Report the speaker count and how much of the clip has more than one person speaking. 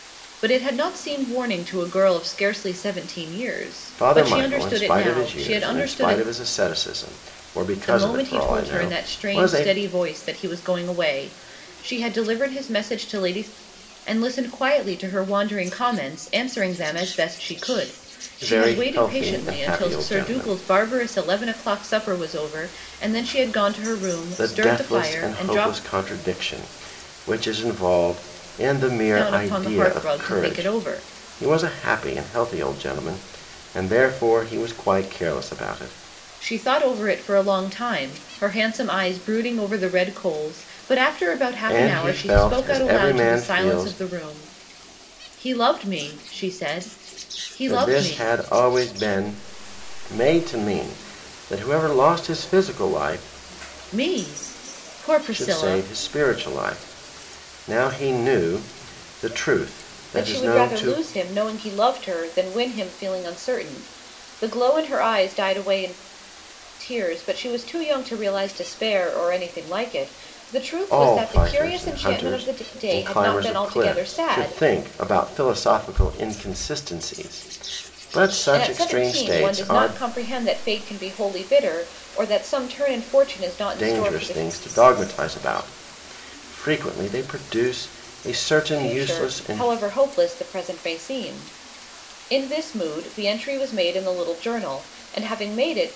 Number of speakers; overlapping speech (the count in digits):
2, about 22%